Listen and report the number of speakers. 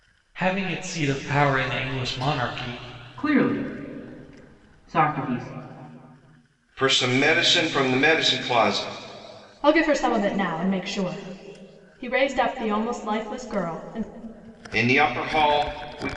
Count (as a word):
four